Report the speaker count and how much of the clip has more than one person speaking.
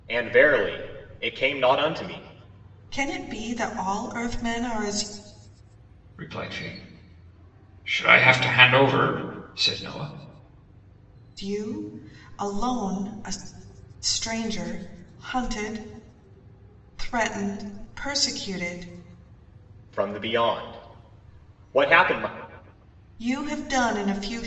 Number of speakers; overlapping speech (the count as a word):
three, no overlap